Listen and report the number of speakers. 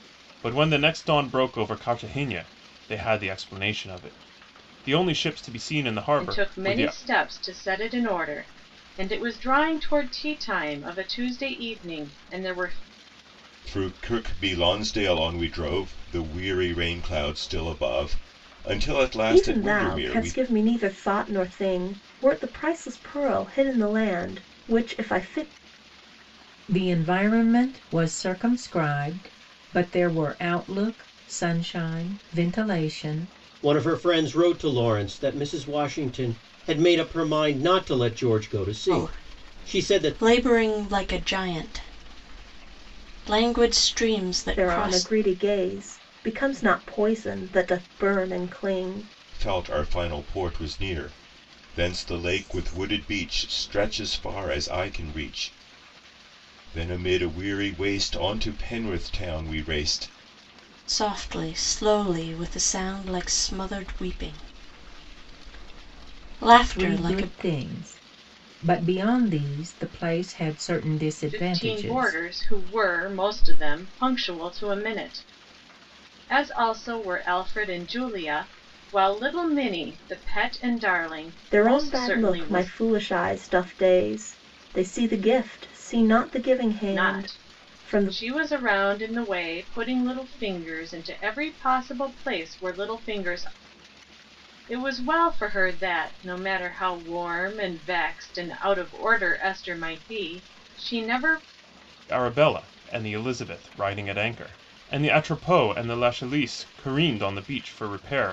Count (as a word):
seven